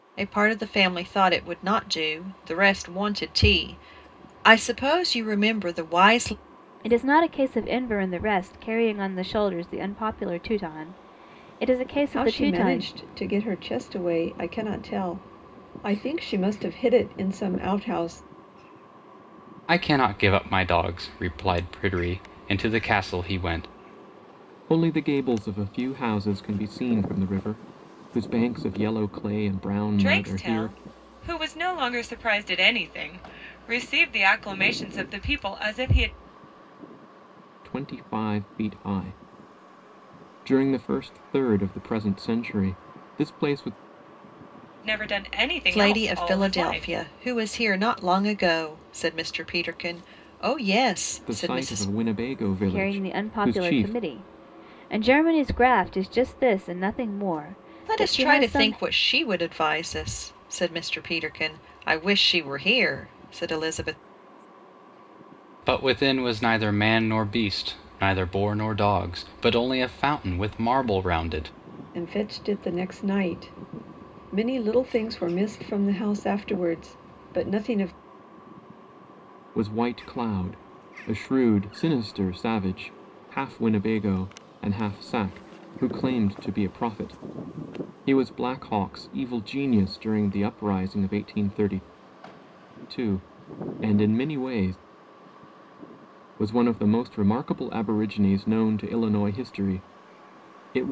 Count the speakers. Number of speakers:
six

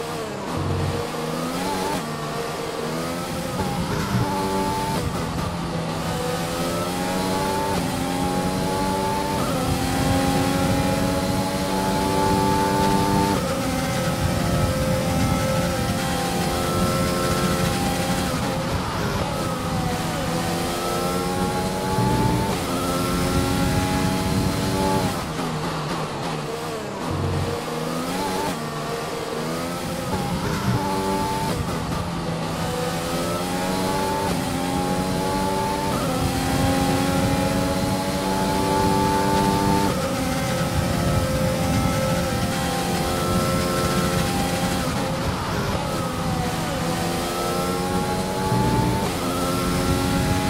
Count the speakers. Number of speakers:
zero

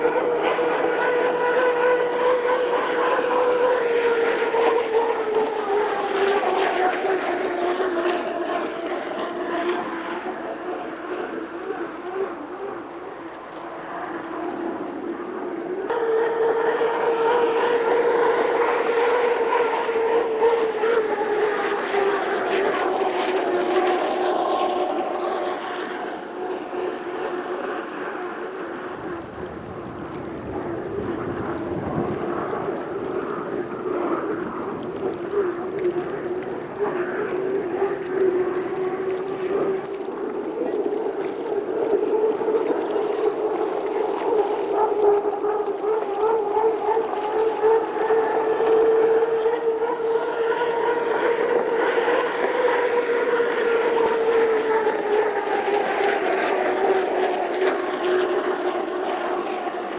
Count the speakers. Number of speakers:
zero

